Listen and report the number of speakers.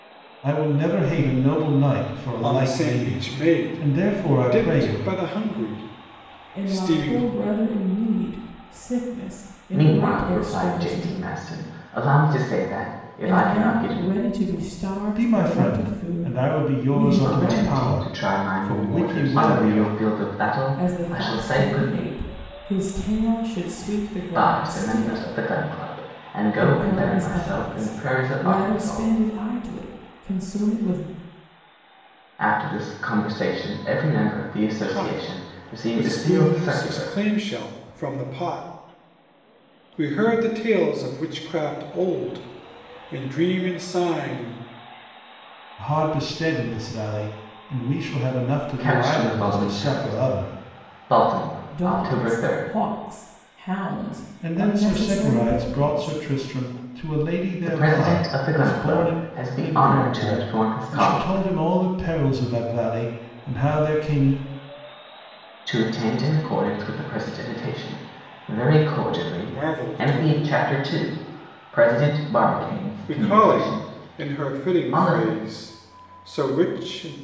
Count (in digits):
4